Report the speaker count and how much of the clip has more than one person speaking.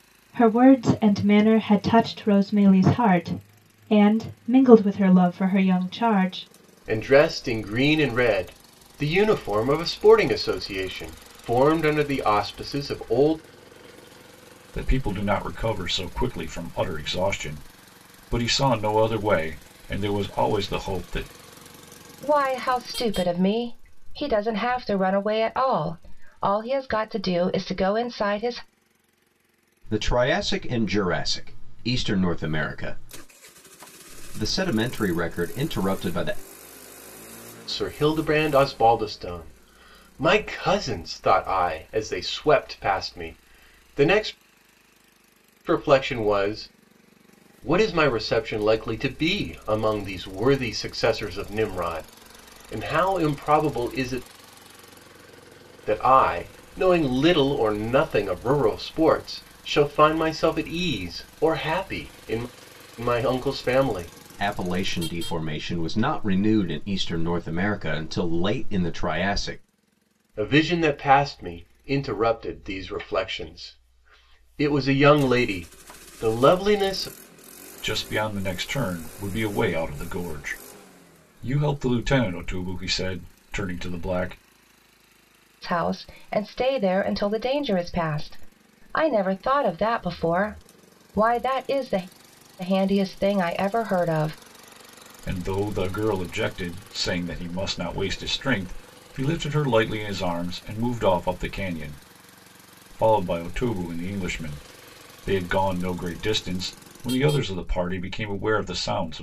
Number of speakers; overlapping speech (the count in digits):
5, no overlap